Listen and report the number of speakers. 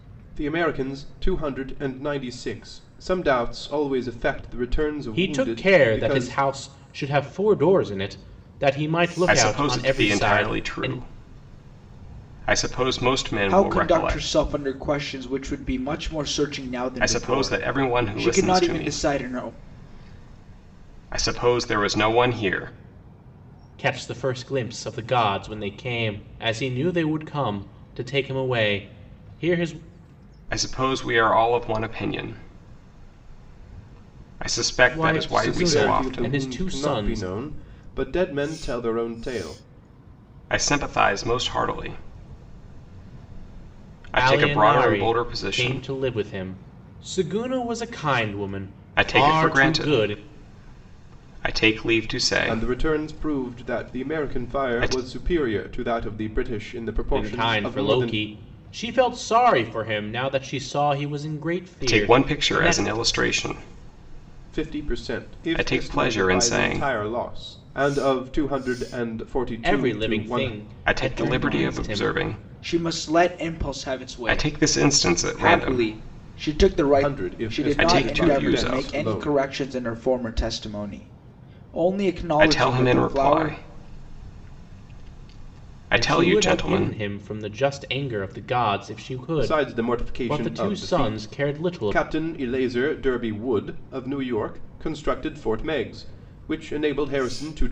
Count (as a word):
four